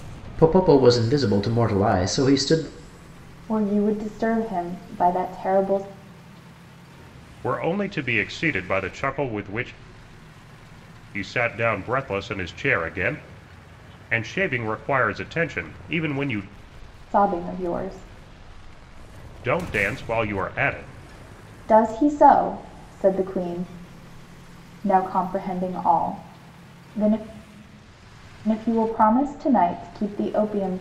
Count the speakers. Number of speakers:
three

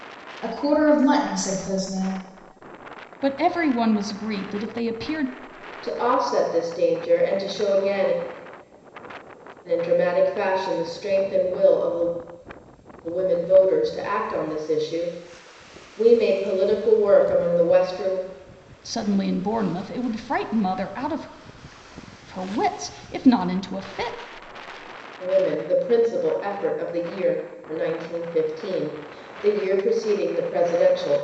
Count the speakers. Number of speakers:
three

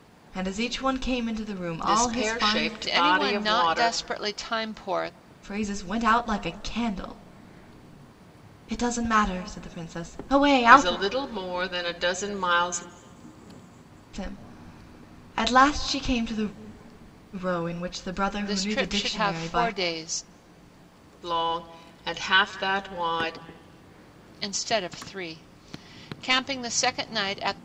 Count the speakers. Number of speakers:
three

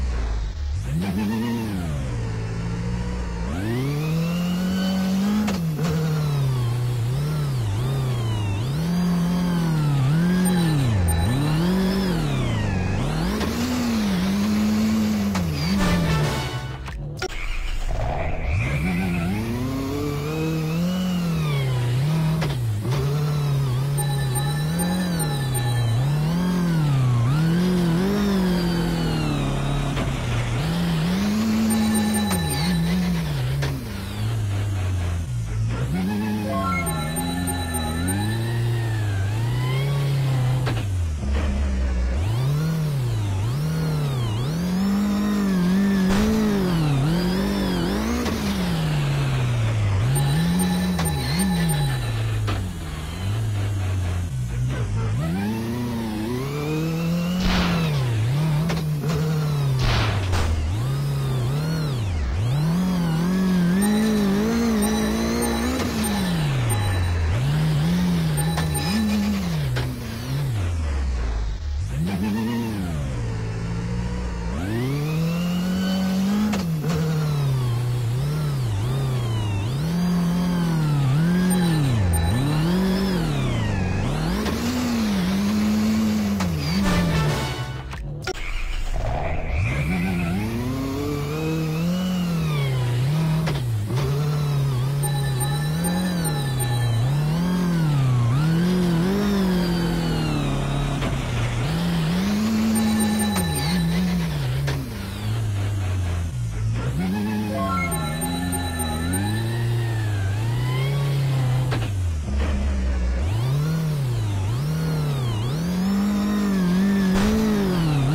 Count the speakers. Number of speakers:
zero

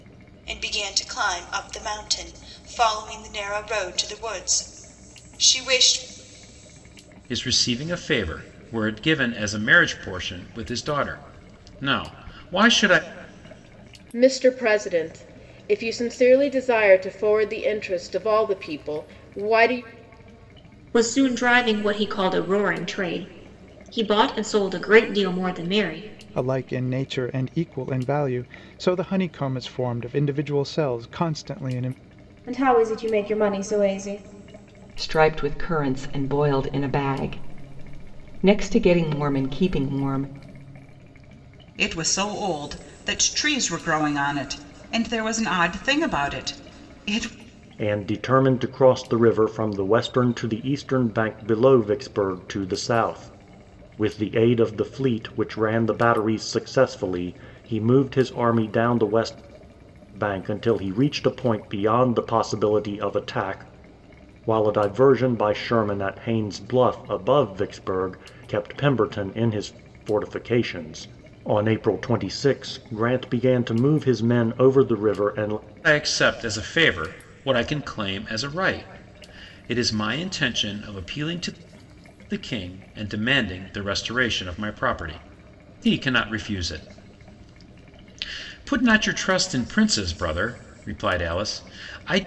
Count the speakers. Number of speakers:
nine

